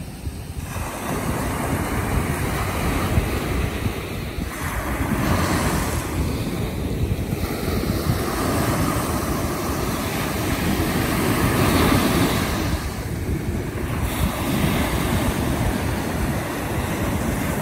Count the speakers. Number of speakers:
0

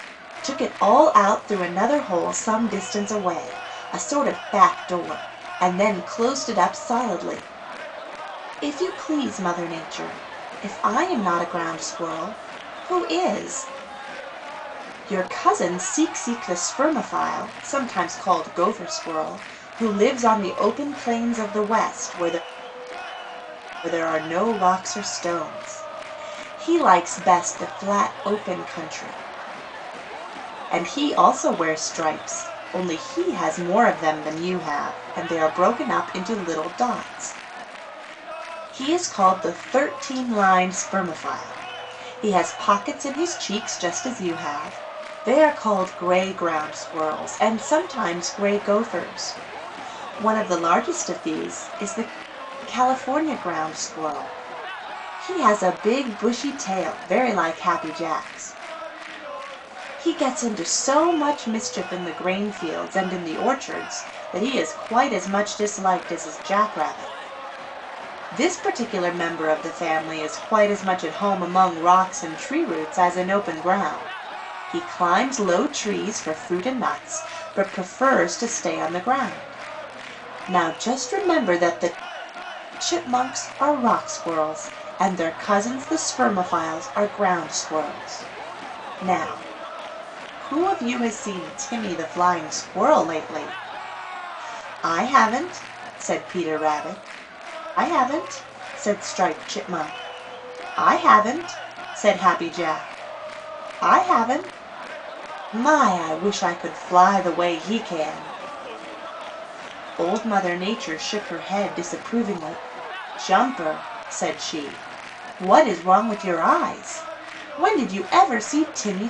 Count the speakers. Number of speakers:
1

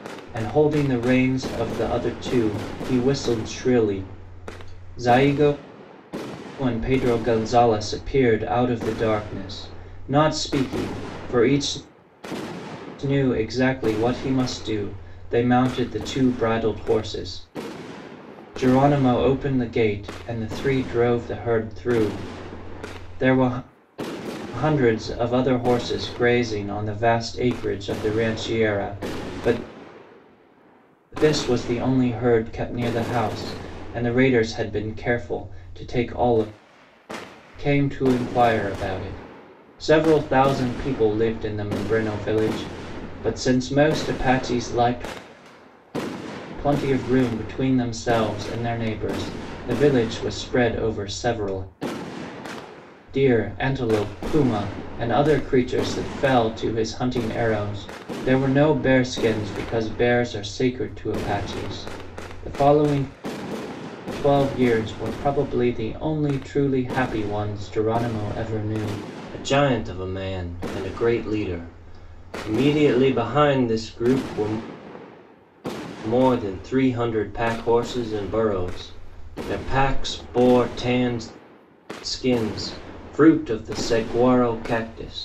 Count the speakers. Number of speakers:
1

